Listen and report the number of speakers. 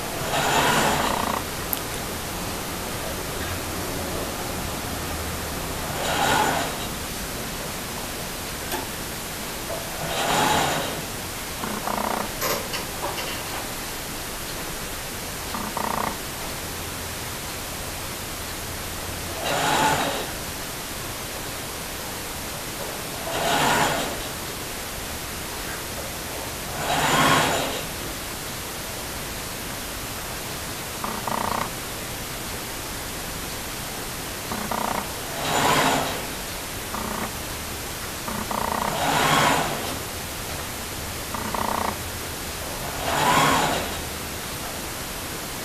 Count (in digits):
0